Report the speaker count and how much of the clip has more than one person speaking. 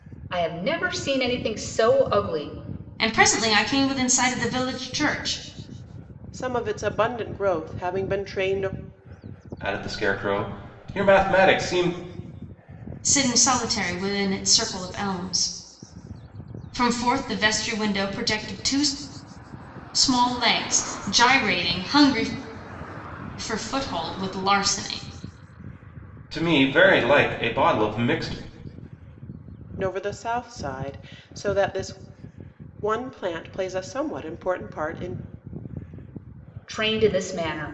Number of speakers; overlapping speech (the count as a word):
four, no overlap